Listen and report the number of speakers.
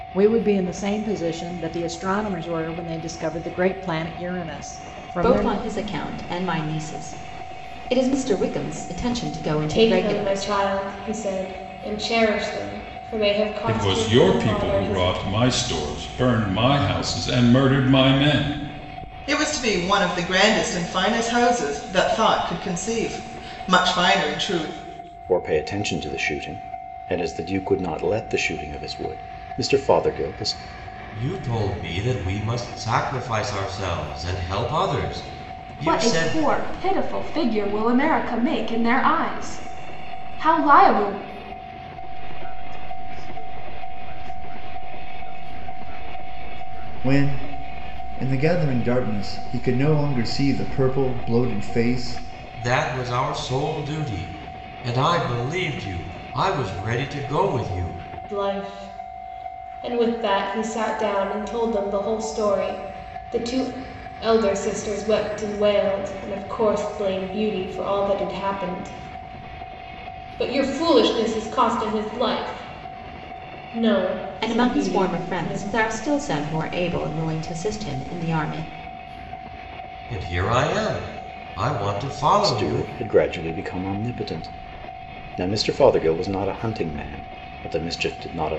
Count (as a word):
ten